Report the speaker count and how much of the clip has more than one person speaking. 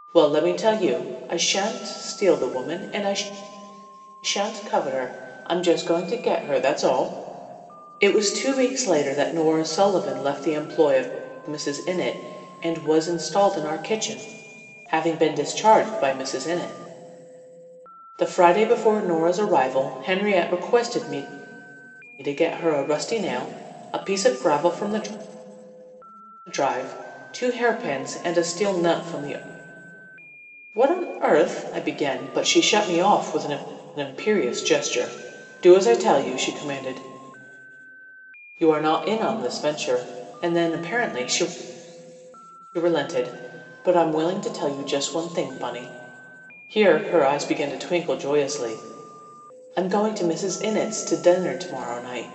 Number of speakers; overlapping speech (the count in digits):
1, no overlap